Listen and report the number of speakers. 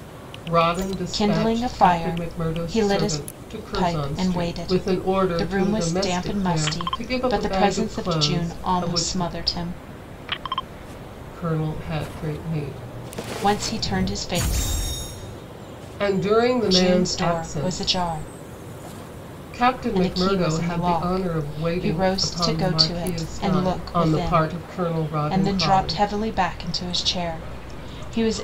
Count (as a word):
two